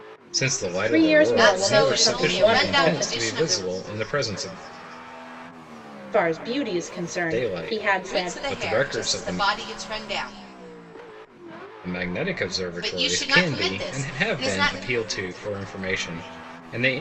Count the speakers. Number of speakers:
3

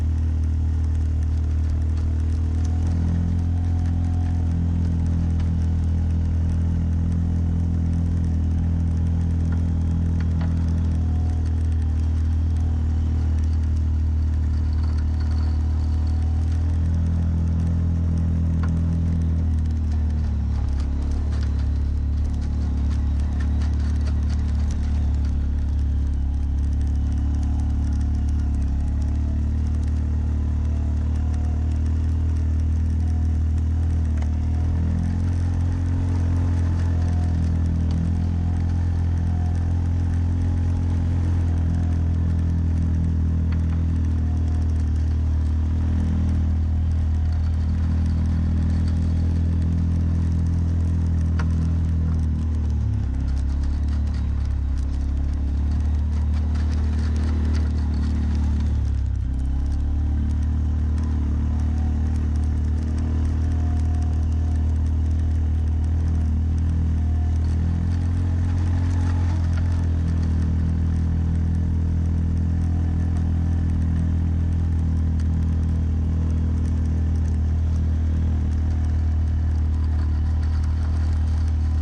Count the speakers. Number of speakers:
0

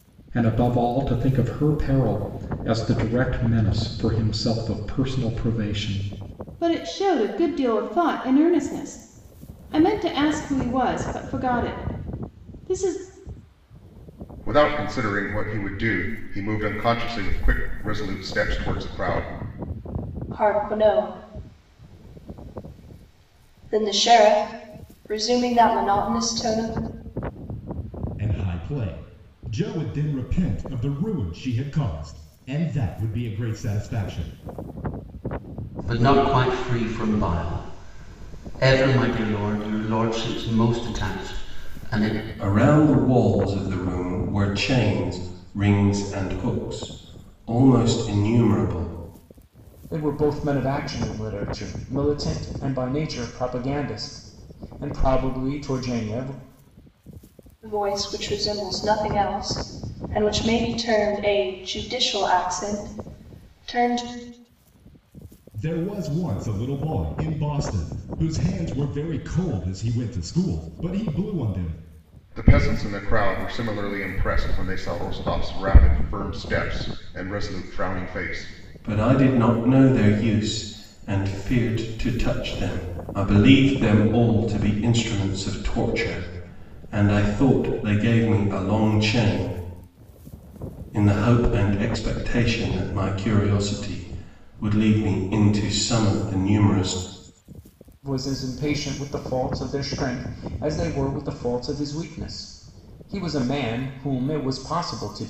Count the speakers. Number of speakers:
8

